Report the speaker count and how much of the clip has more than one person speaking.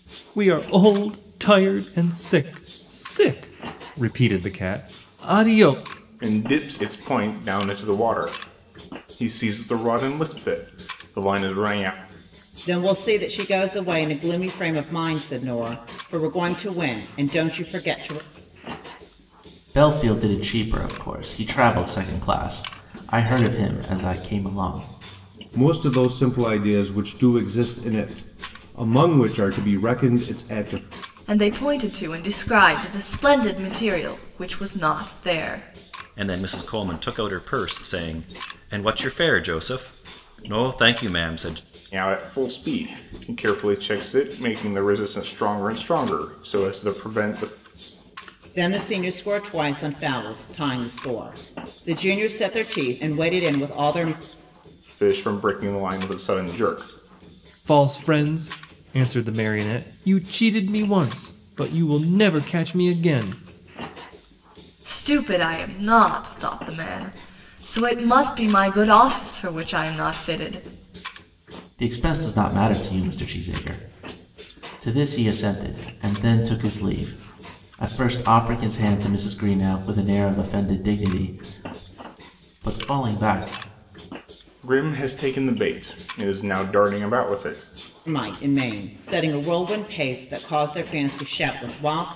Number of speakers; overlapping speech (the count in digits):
7, no overlap